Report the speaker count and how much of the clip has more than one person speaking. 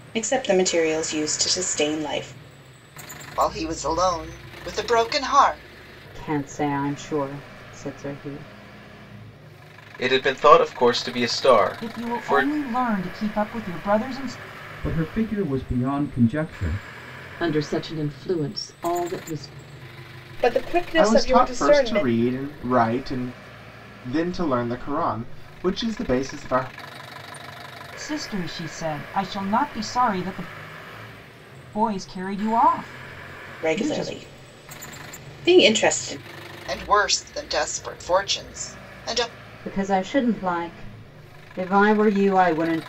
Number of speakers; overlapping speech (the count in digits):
9, about 6%